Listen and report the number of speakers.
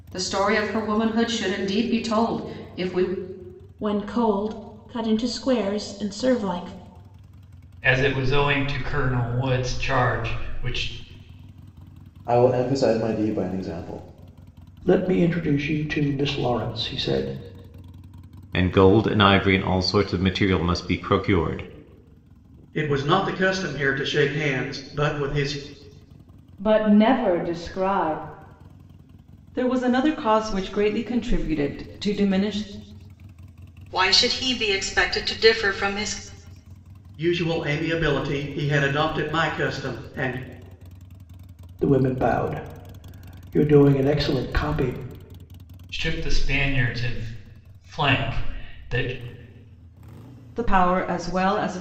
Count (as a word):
ten